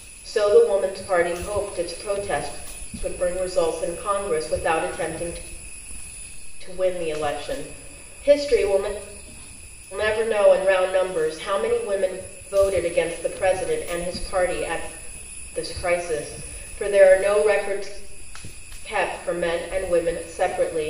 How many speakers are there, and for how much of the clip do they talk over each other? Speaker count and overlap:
1, no overlap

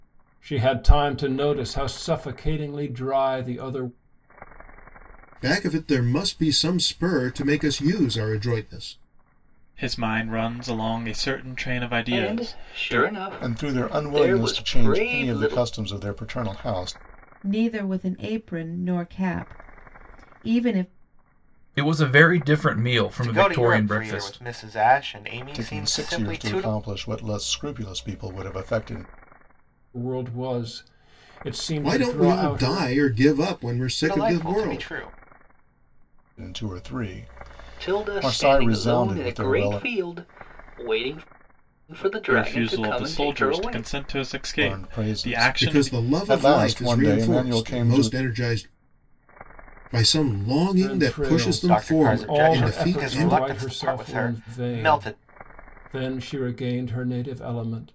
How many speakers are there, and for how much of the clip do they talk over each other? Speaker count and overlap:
8, about 33%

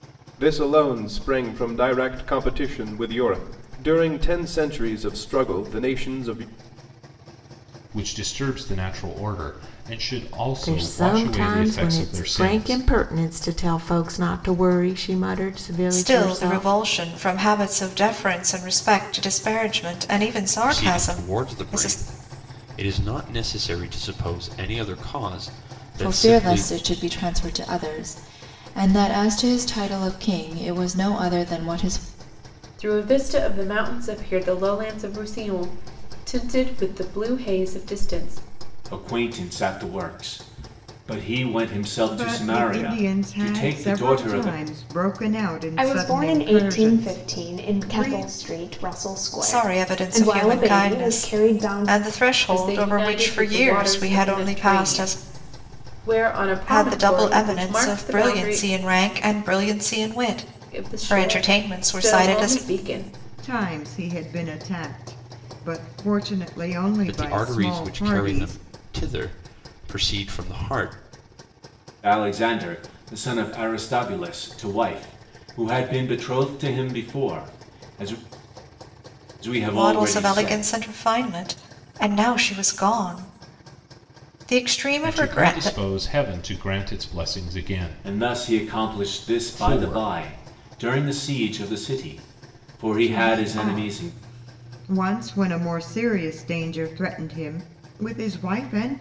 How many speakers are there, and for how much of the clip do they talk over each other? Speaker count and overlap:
10, about 26%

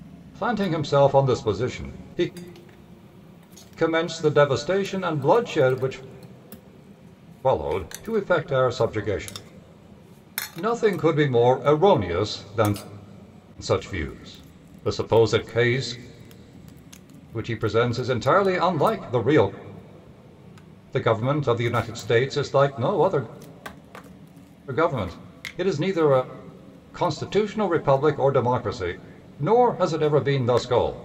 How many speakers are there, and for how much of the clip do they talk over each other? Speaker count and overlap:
1, no overlap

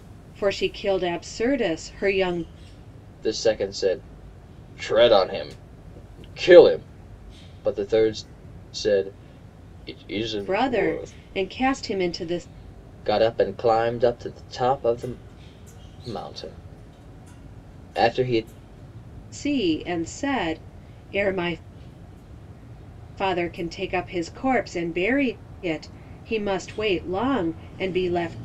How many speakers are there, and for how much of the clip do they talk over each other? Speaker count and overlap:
2, about 3%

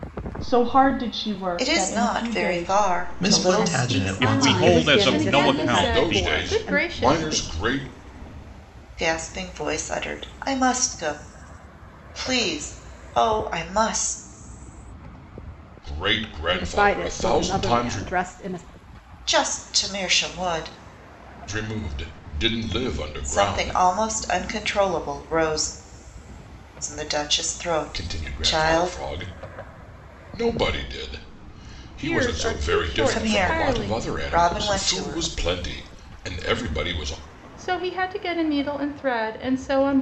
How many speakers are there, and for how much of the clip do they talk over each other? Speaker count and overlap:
8, about 30%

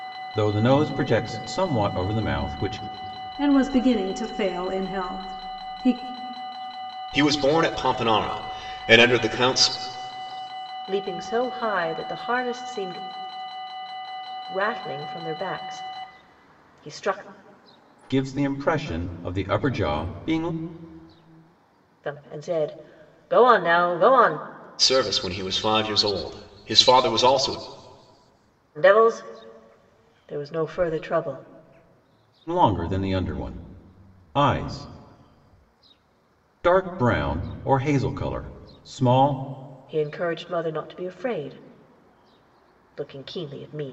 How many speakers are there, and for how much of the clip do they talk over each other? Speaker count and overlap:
4, no overlap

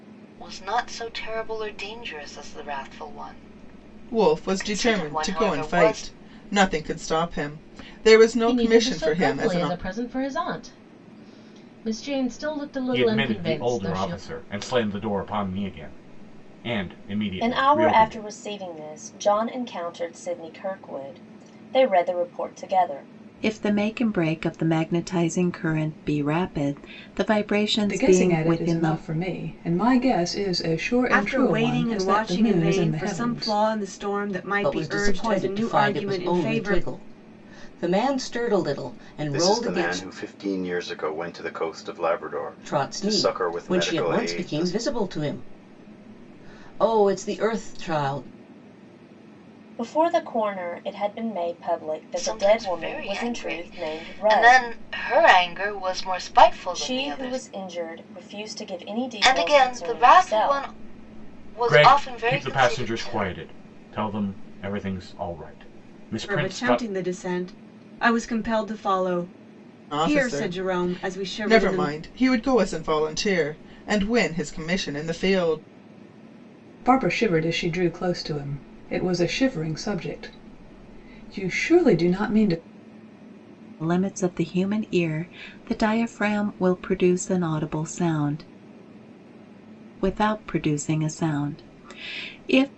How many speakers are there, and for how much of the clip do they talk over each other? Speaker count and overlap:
10, about 26%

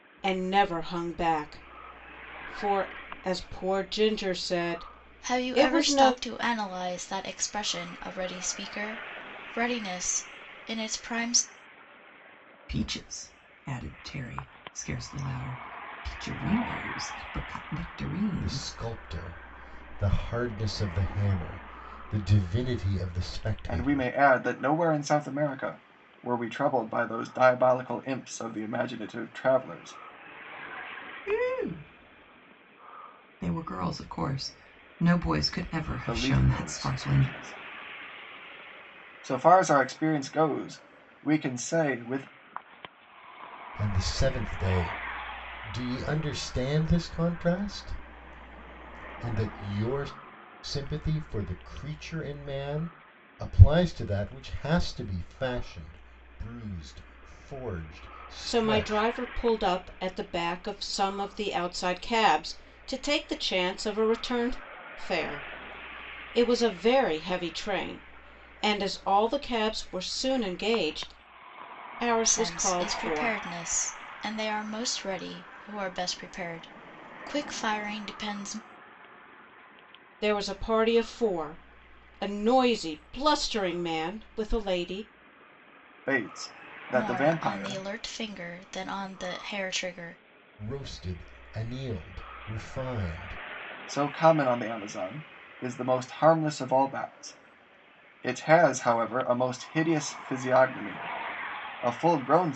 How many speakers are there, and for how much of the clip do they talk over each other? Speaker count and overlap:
5, about 6%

